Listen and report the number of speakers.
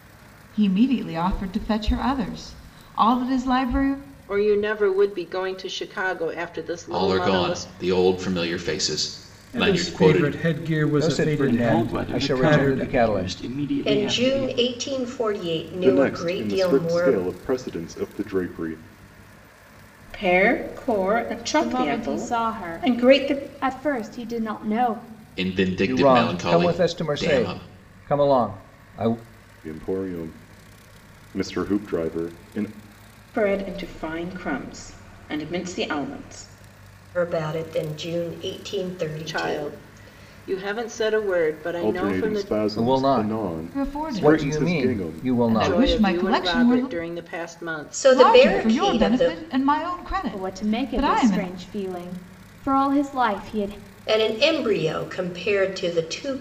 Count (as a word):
ten